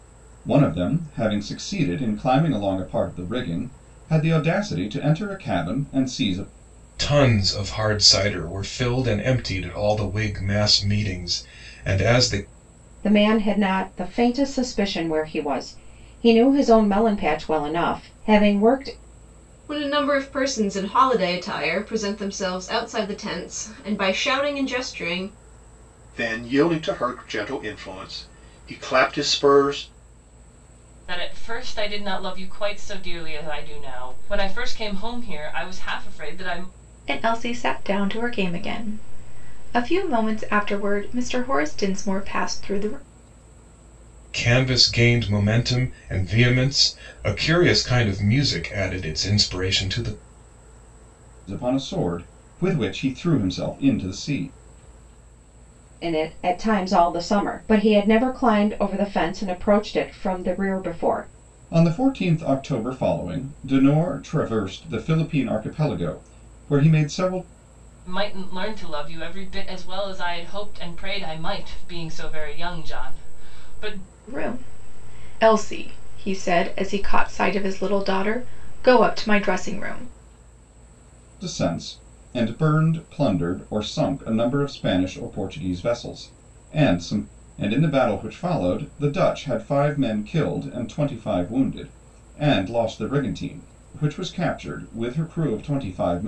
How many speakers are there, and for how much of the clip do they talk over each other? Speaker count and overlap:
7, no overlap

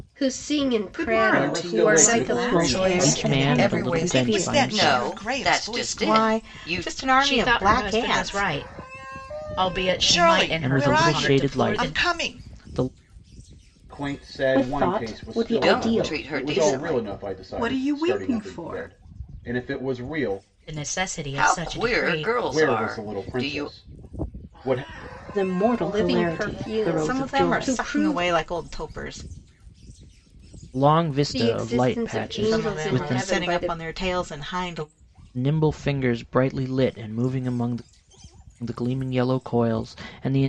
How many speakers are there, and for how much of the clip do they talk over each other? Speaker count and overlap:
10, about 52%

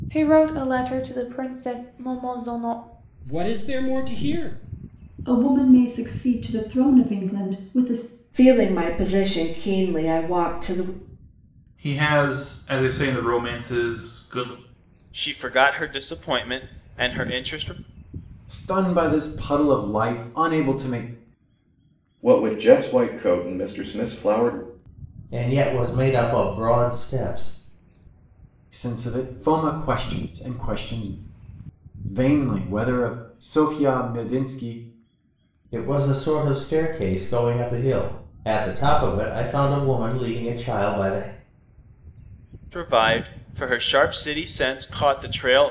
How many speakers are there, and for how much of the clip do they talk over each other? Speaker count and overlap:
9, no overlap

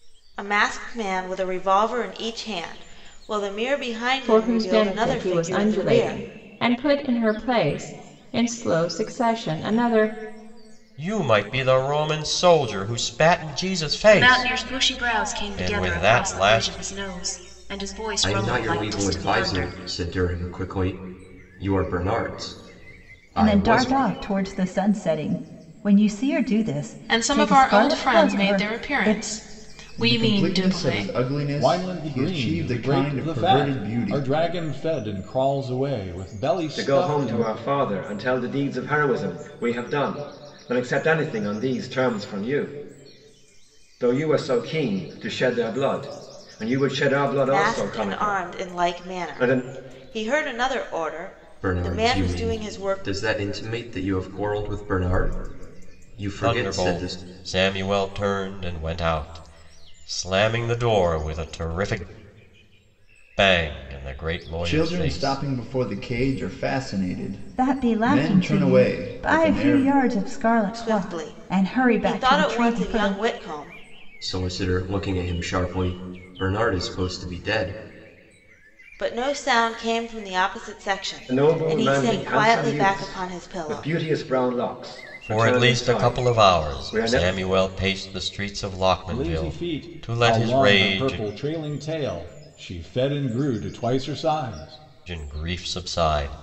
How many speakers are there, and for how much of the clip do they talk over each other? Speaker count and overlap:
10, about 32%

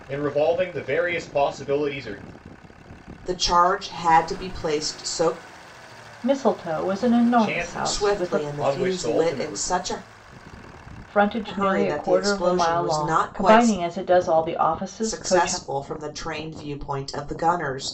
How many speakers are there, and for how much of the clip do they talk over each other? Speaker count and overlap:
3, about 28%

